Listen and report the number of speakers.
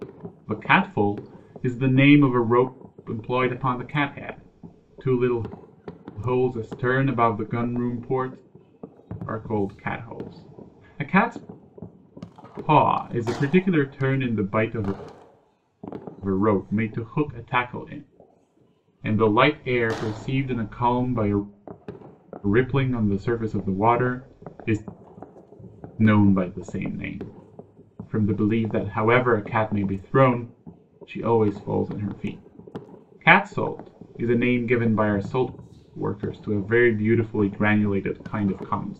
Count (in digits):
1